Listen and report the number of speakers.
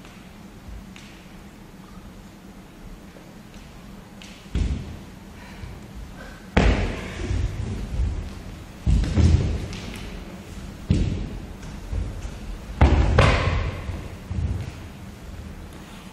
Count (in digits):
0